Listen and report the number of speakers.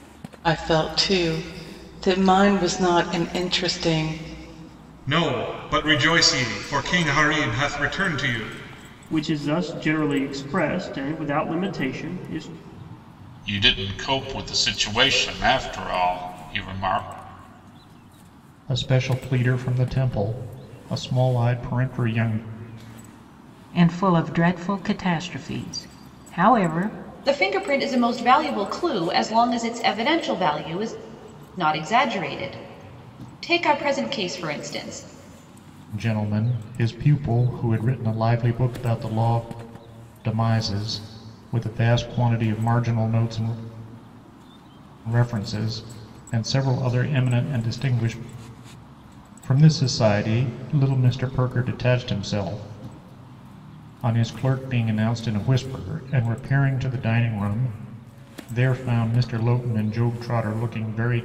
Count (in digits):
7